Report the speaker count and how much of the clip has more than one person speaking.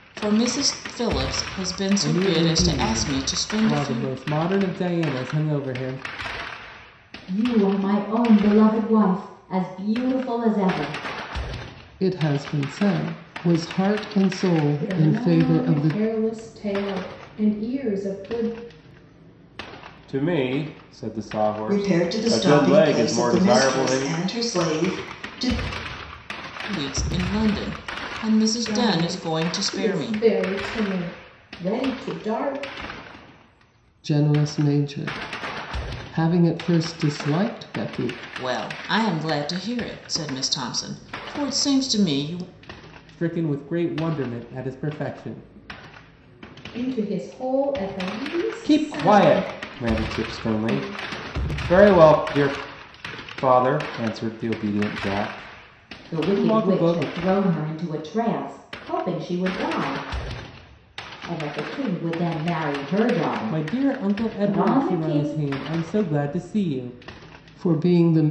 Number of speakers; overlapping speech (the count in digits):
7, about 19%